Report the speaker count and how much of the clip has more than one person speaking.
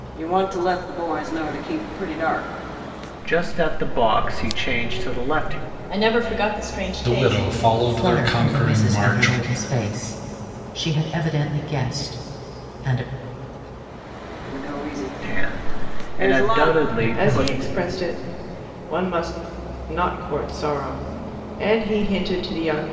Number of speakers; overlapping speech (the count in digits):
5, about 19%